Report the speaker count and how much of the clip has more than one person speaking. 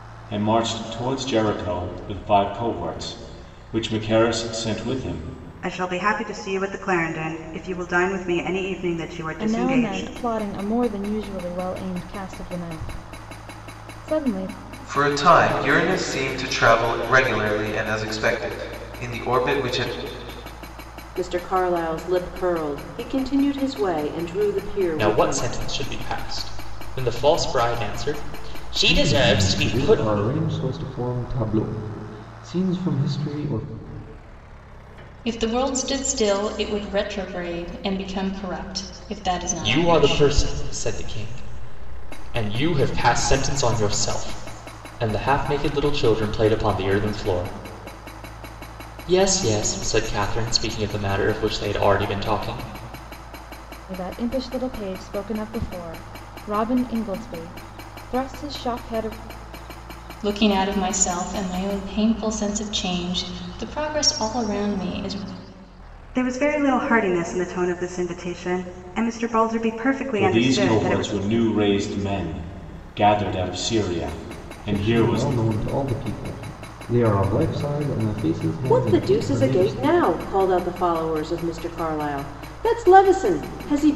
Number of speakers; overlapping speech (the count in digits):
8, about 7%